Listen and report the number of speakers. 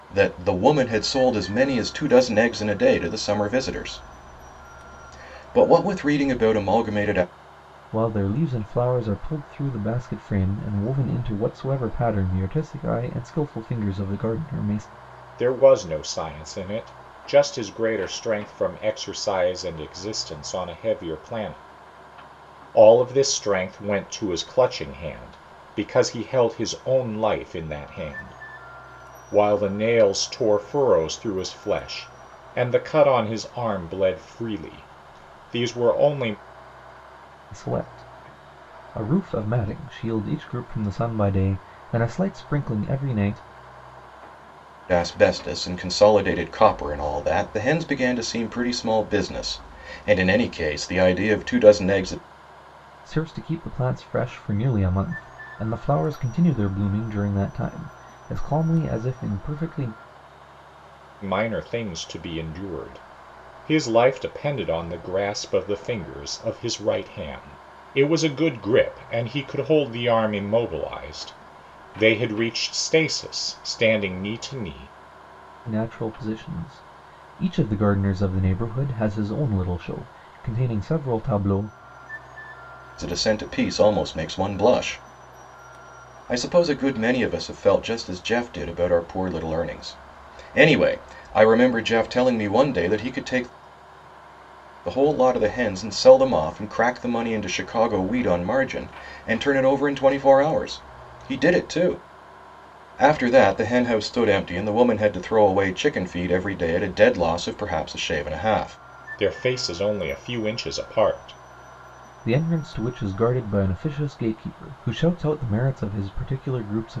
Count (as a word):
three